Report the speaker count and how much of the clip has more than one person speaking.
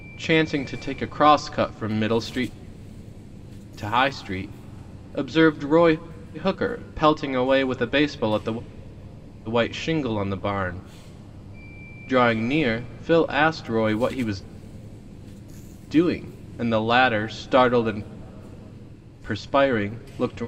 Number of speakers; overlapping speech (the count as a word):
one, no overlap